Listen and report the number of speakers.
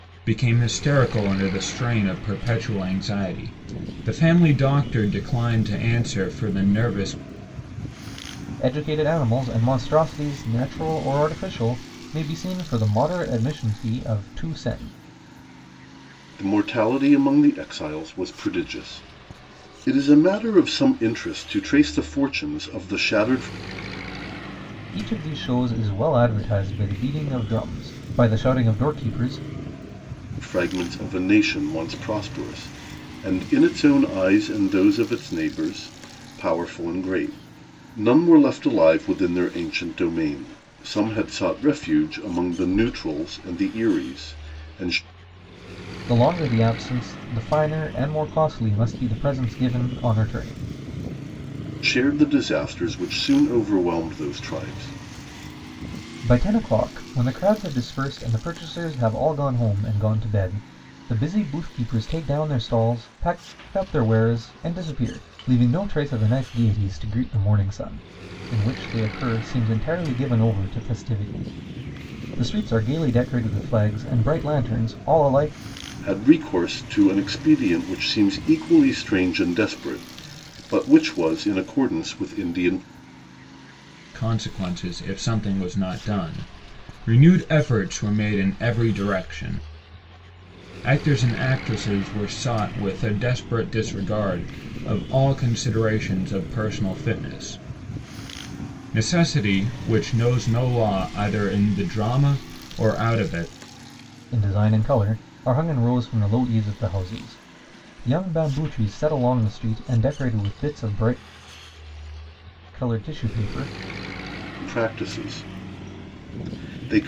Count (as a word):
three